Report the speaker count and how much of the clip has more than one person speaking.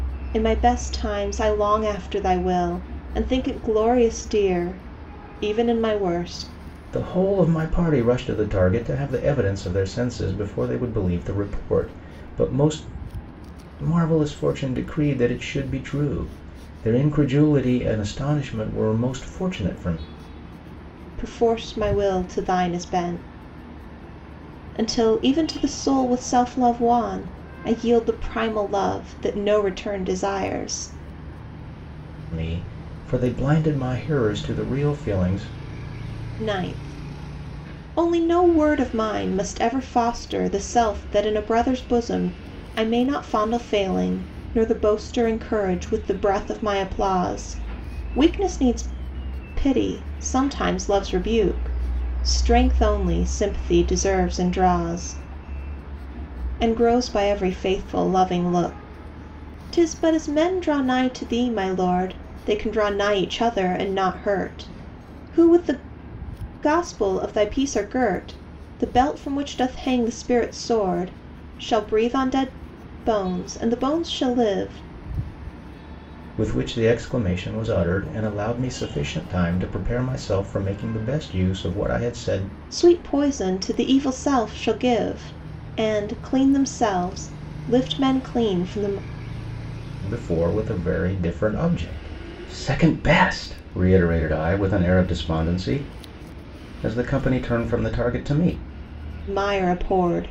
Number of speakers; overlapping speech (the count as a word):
two, no overlap